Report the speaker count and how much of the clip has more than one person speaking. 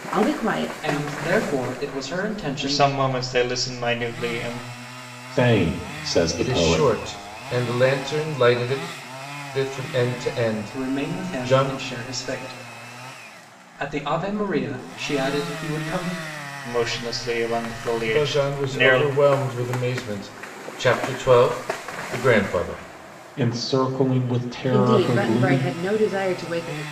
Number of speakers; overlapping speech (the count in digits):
5, about 18%